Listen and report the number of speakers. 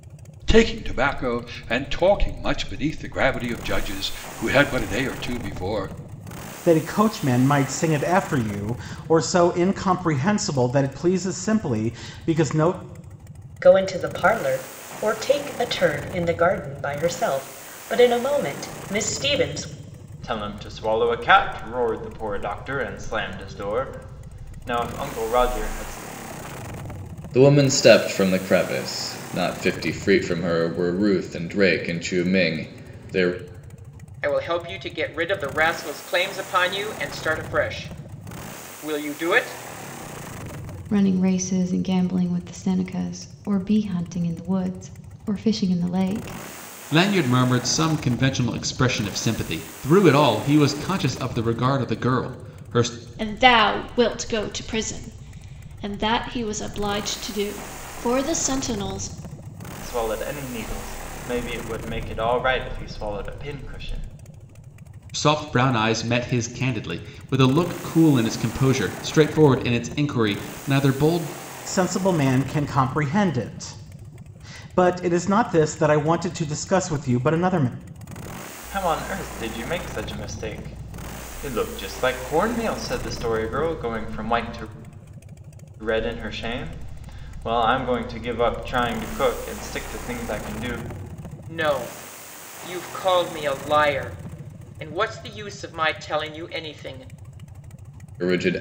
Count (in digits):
9